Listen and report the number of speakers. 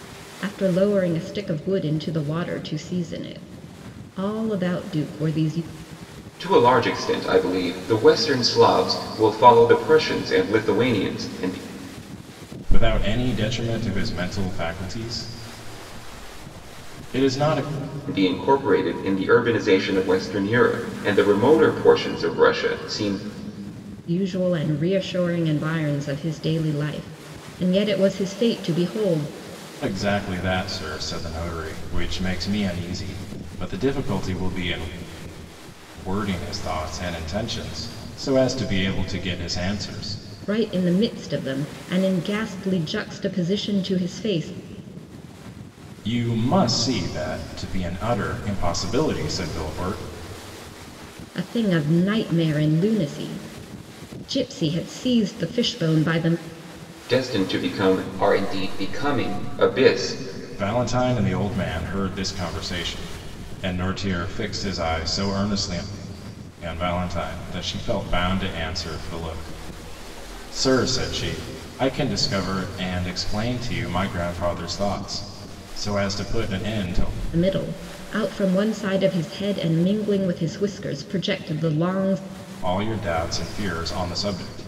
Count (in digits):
3